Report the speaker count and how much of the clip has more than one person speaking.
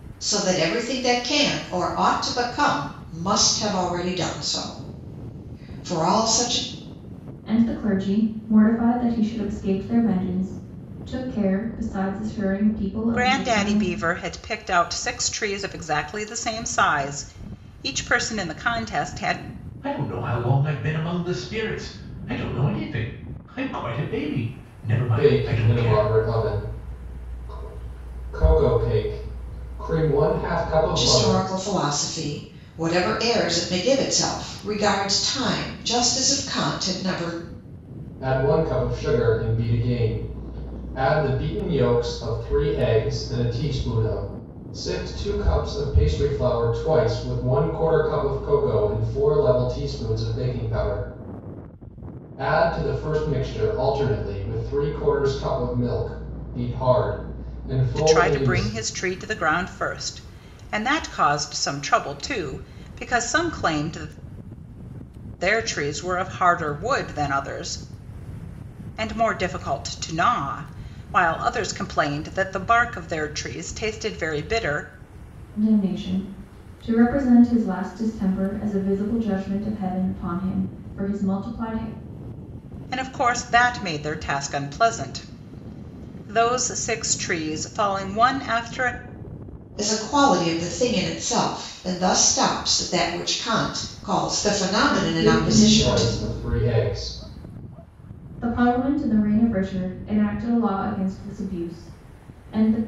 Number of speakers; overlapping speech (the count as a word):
five, about 5%